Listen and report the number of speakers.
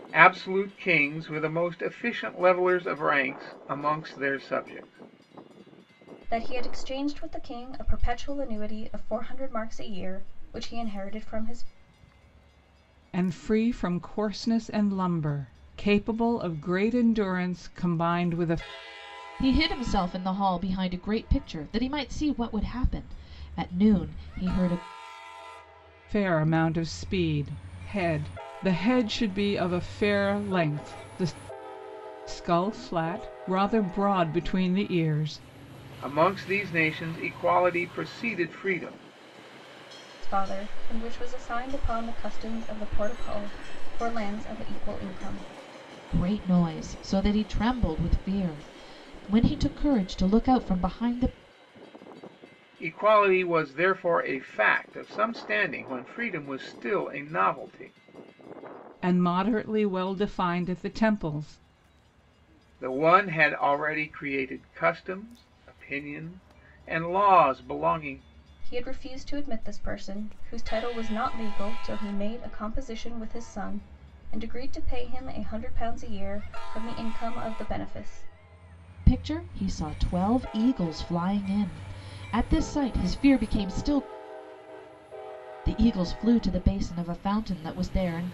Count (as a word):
four